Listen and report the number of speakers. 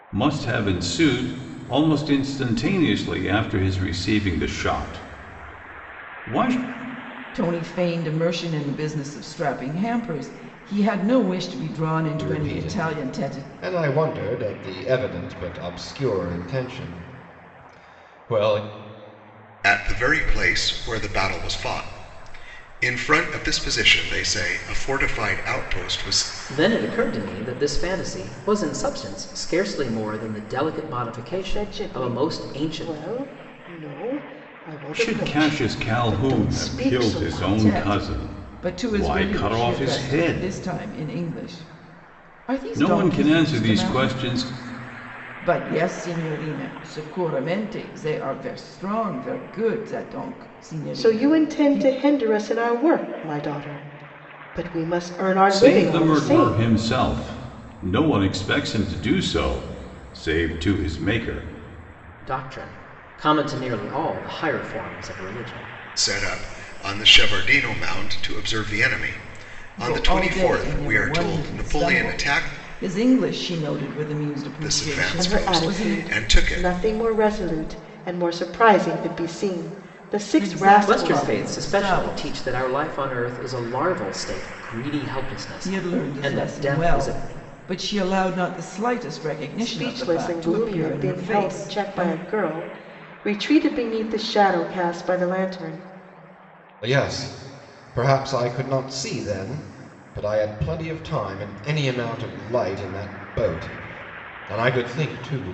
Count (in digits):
6